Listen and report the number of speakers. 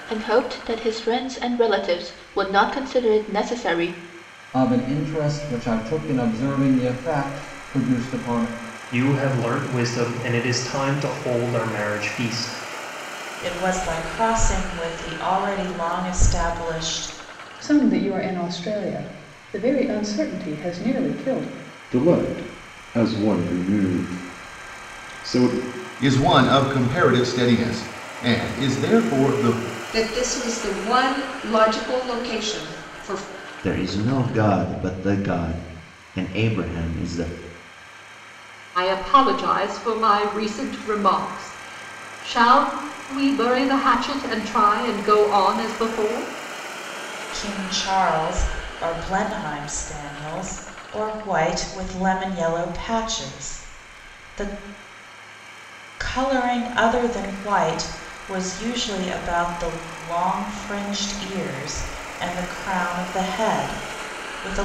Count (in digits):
10